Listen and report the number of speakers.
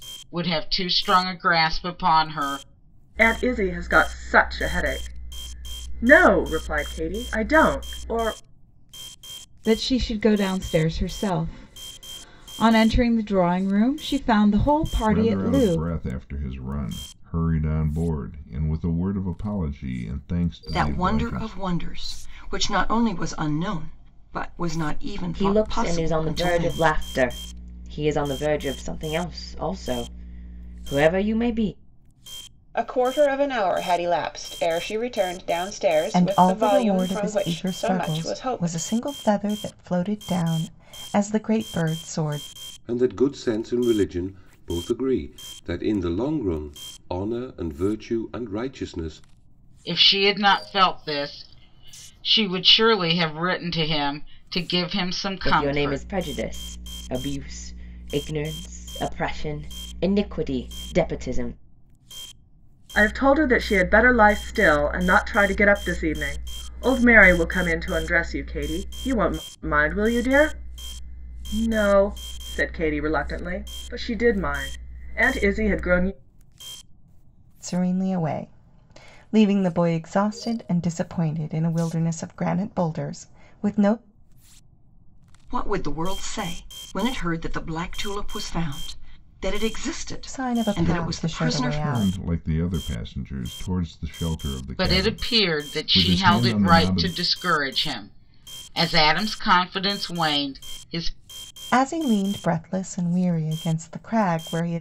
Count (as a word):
nine